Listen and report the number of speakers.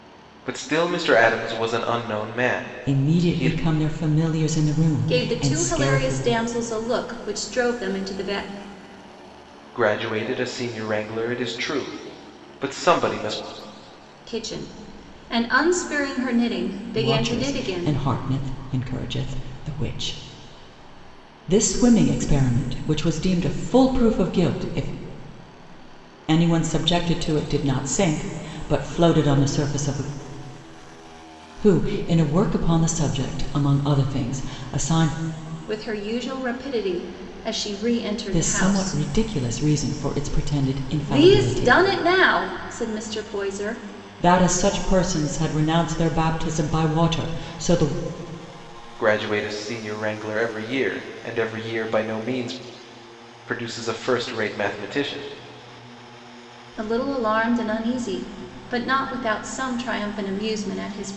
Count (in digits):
3